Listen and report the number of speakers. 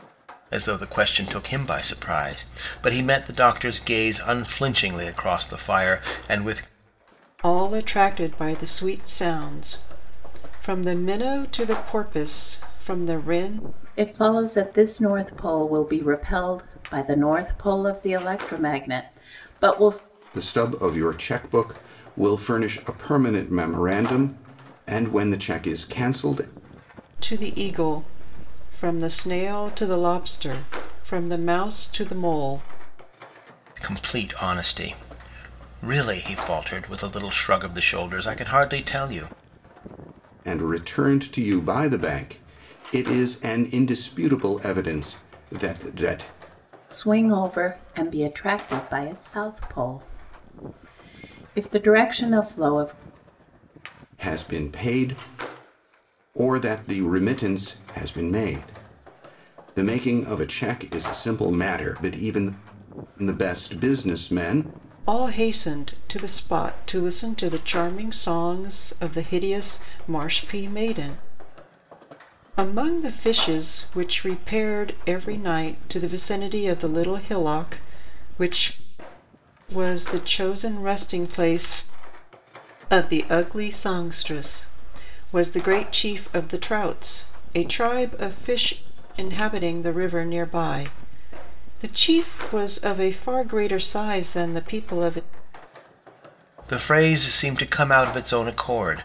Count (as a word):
four